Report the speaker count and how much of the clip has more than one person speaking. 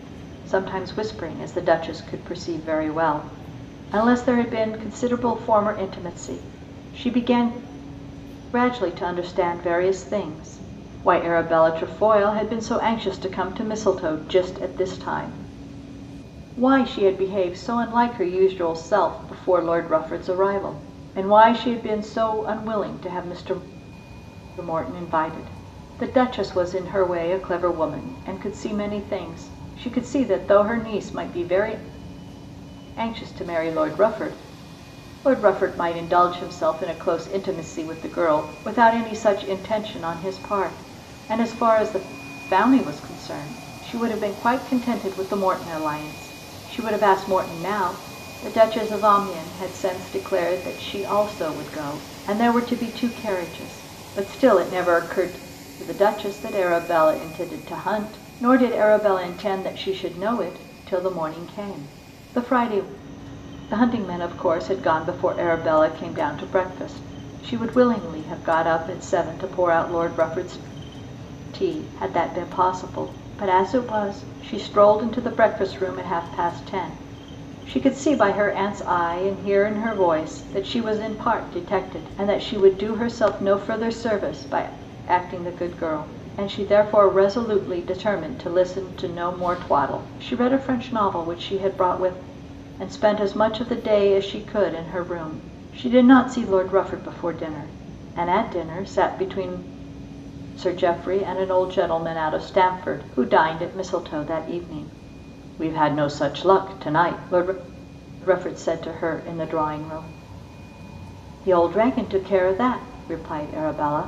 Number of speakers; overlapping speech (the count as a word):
one, no overlap